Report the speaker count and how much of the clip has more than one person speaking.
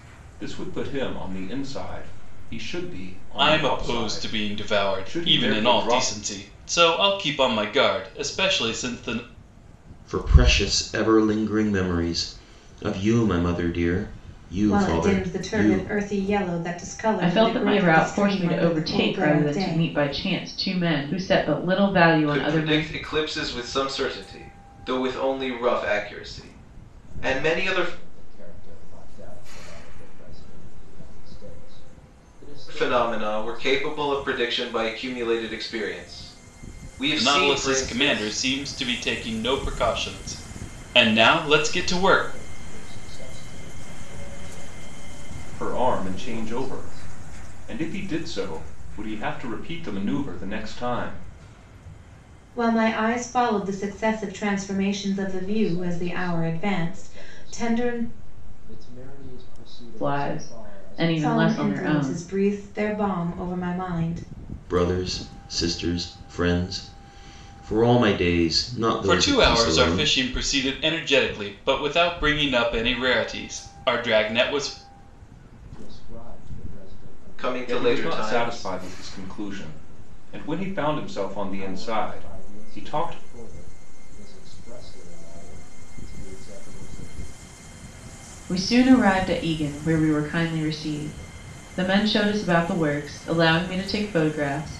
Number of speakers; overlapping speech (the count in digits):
7, about 24%